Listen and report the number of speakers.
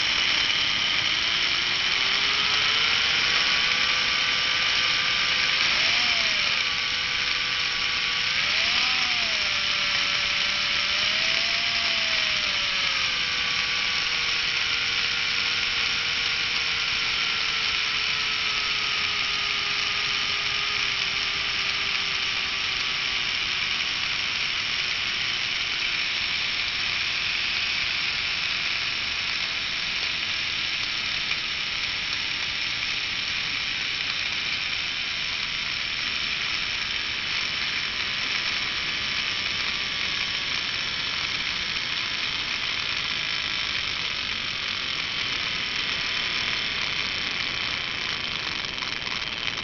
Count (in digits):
0